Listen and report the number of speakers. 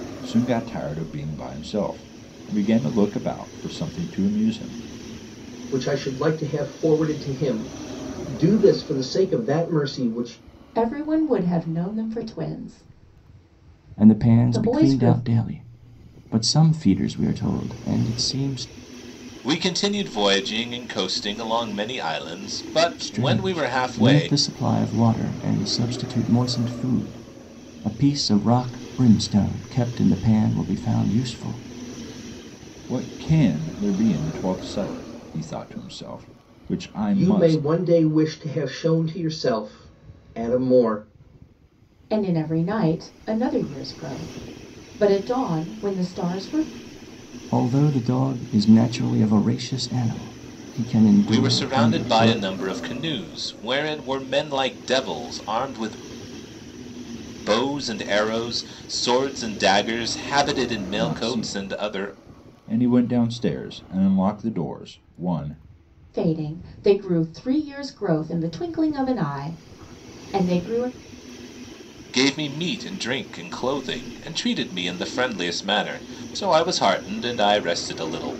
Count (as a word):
five